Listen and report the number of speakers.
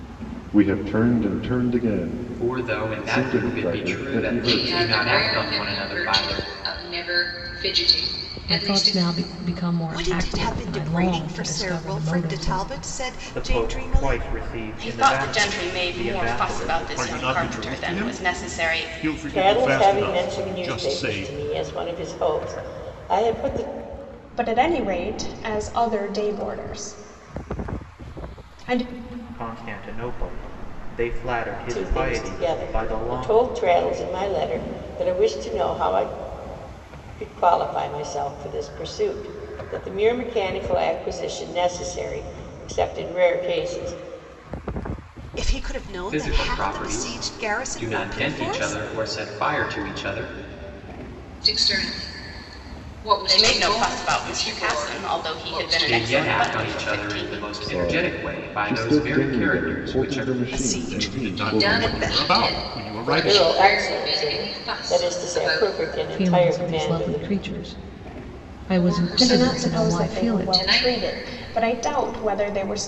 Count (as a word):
ten